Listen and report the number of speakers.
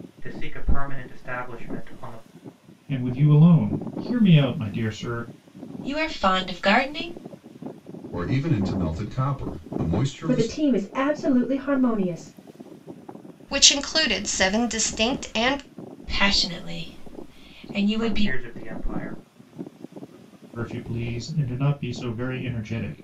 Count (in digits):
6